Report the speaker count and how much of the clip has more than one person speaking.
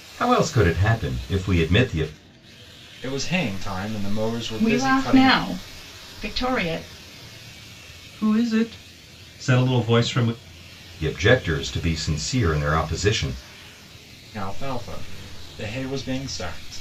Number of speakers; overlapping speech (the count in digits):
4, about 4%